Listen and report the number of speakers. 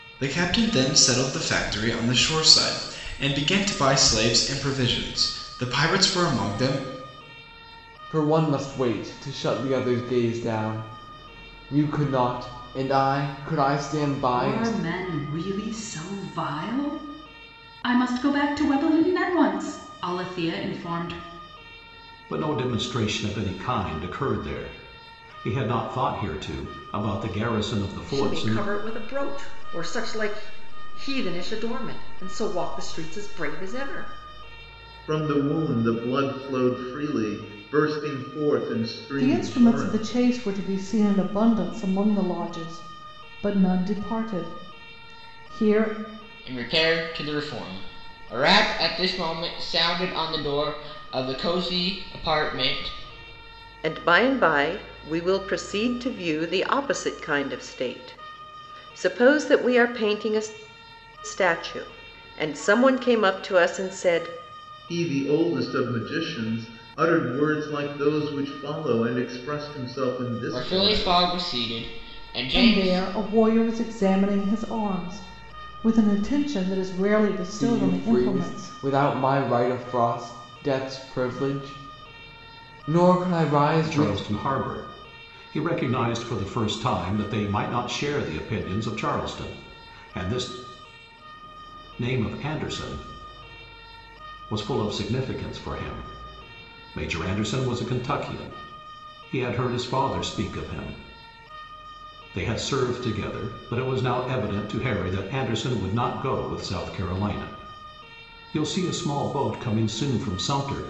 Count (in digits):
9